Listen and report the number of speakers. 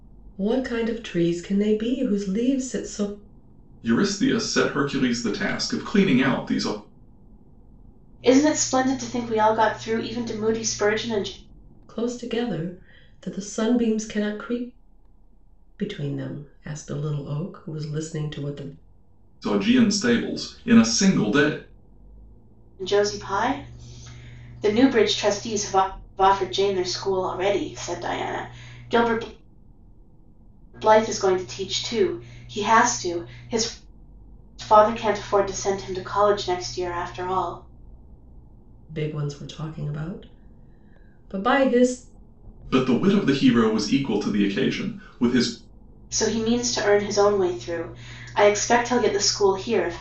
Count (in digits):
3